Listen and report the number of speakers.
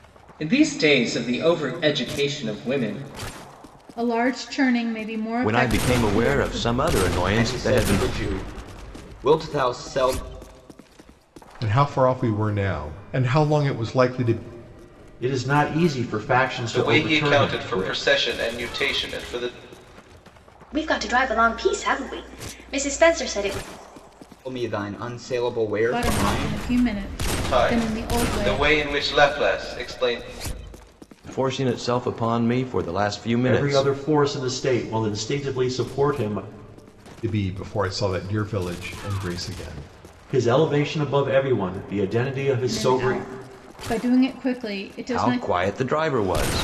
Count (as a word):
eight